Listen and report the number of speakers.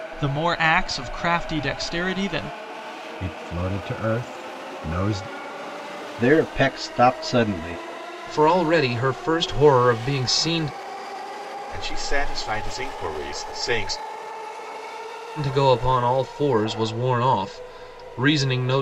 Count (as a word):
five